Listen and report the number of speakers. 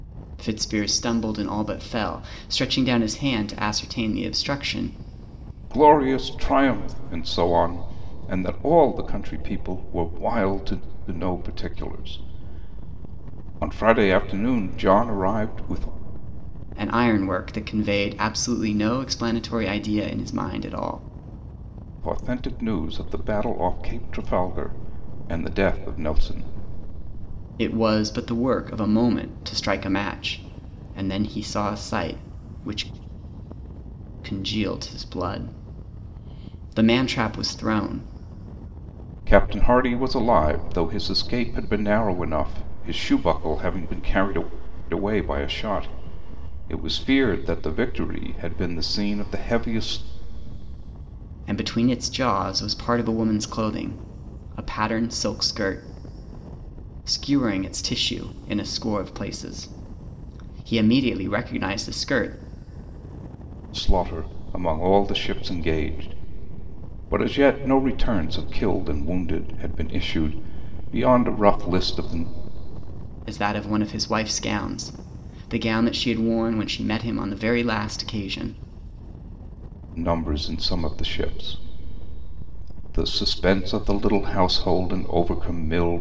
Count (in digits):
2